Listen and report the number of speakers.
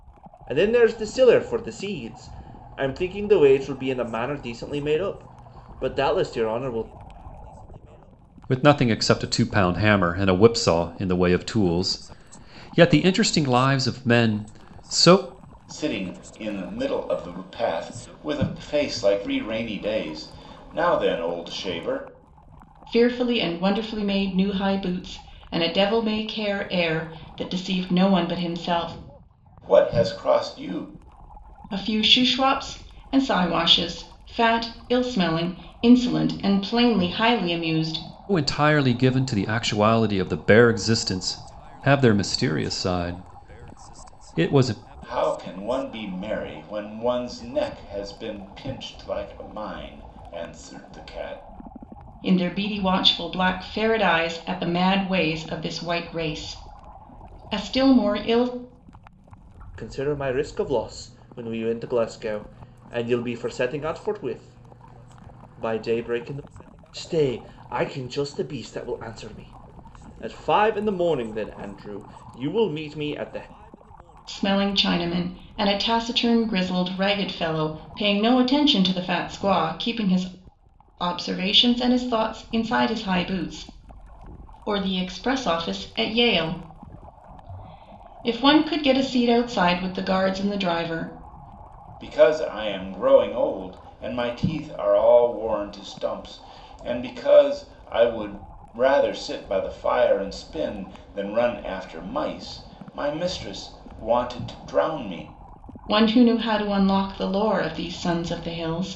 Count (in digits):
4